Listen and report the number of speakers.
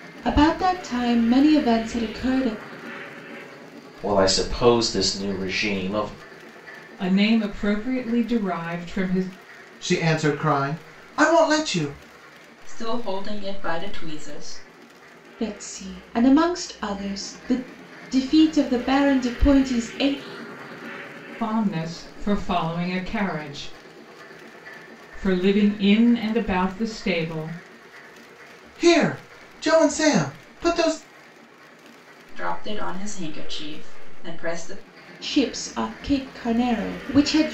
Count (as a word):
five